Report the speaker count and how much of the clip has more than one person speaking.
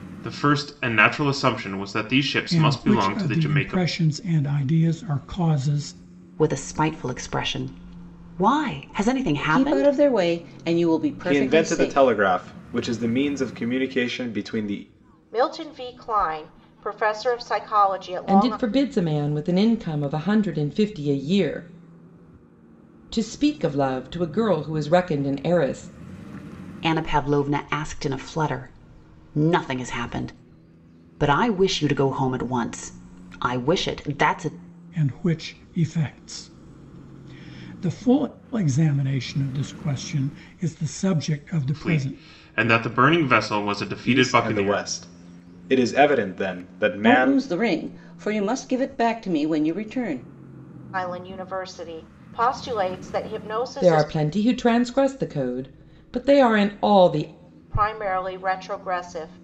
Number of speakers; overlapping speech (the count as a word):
seven, about 9%